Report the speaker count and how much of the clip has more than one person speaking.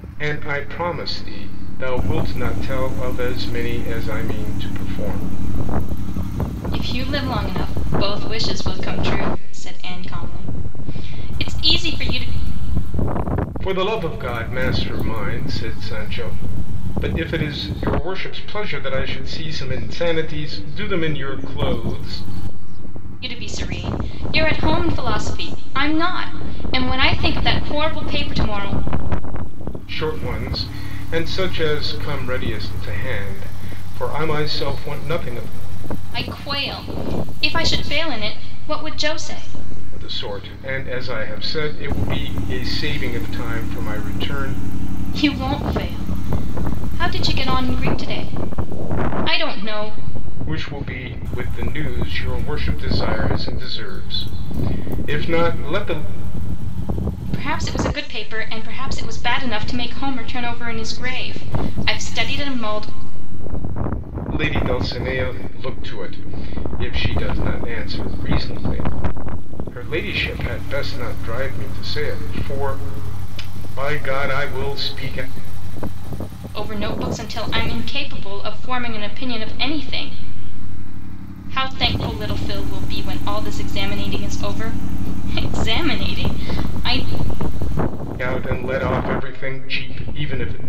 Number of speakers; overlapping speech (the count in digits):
2, no overlap